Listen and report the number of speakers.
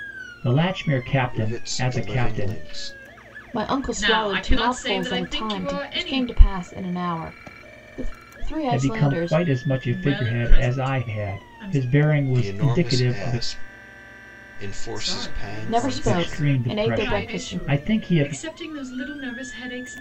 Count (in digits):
4